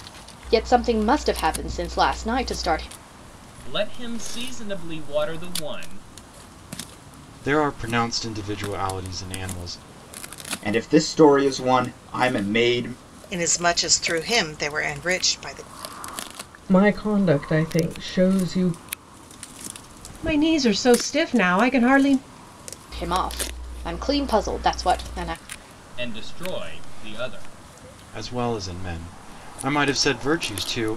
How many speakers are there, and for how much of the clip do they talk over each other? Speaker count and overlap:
seven, no overlap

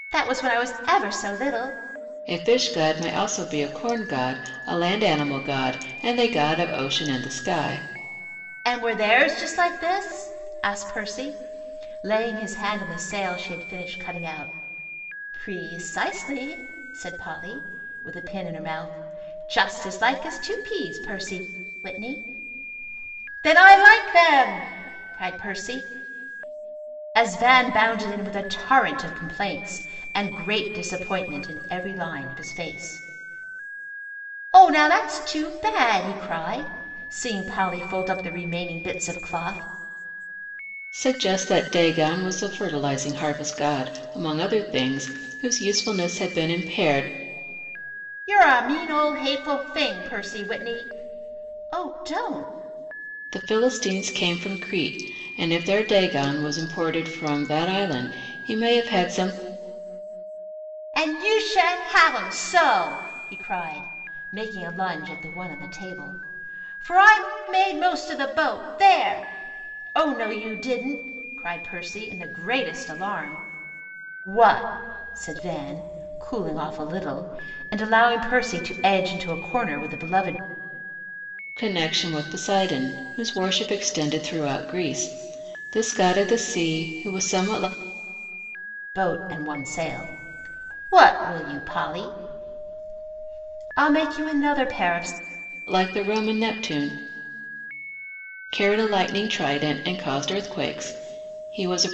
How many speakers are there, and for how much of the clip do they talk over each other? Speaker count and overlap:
two, no overlap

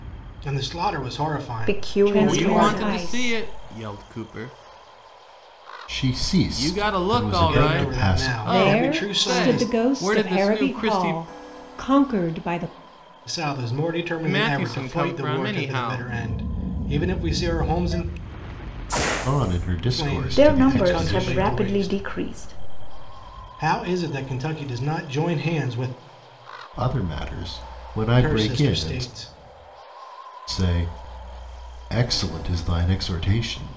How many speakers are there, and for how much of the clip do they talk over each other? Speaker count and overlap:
five, about 34%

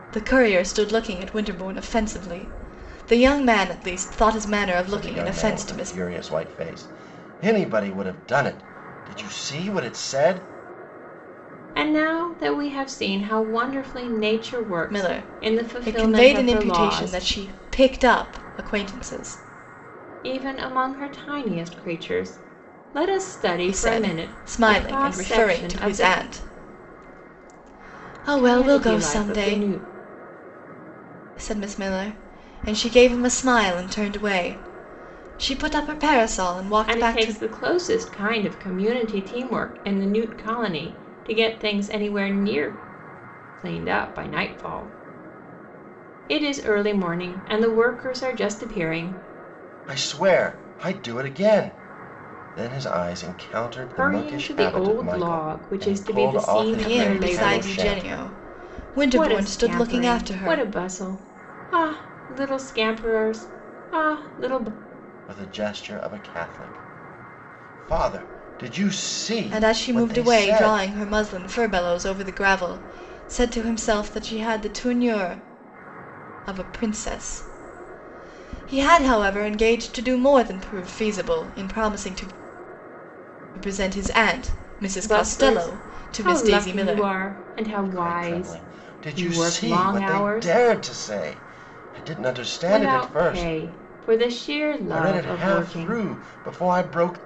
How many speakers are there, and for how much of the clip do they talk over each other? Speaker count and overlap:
three, about 23%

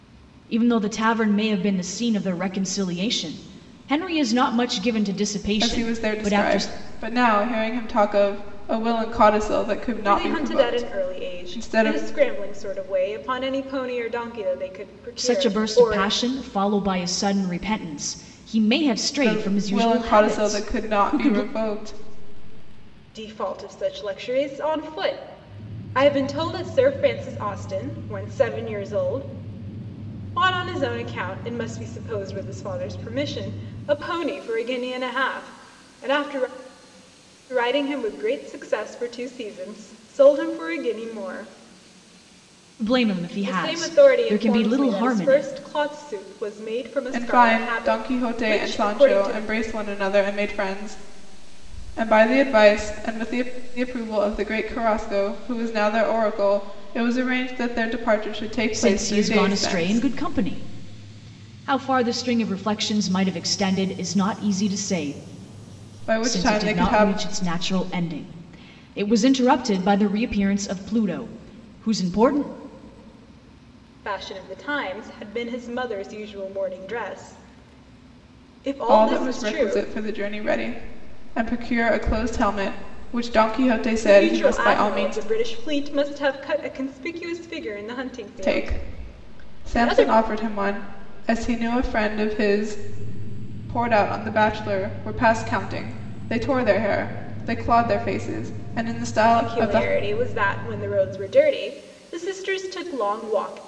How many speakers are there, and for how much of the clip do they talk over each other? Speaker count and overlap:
three, about 17%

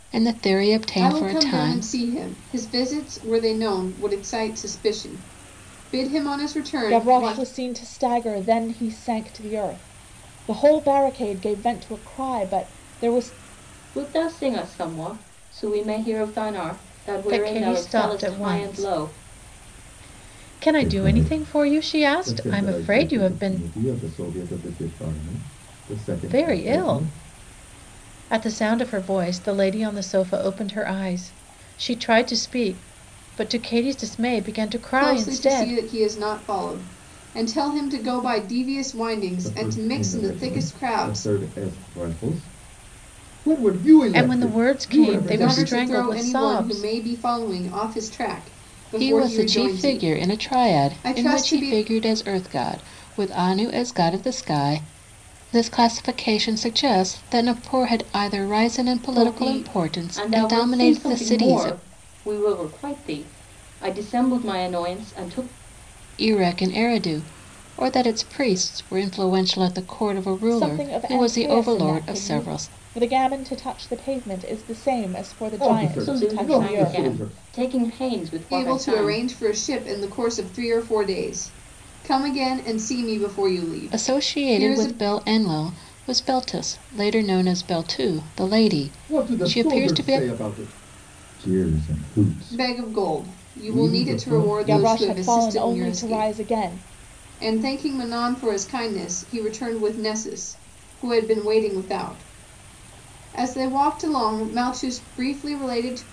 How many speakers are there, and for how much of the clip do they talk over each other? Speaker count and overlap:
six, about 28%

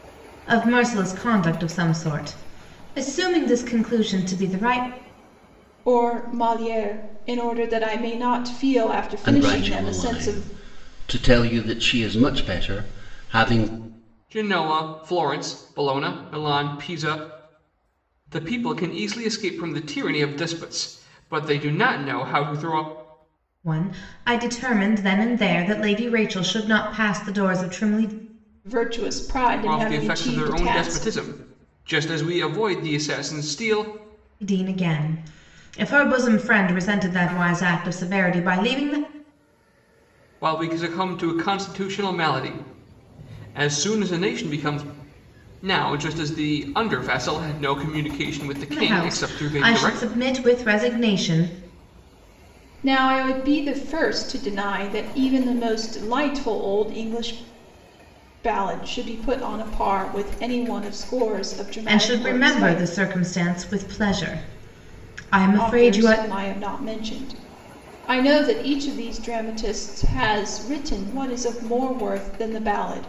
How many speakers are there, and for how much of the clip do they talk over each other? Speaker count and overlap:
four, about 8%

